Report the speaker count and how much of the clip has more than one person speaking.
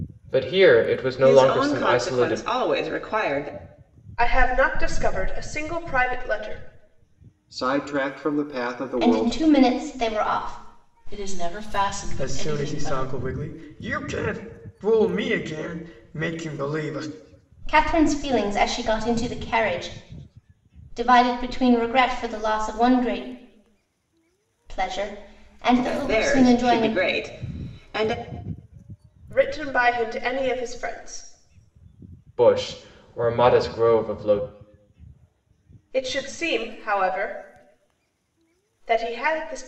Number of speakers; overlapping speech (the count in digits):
7, about 10%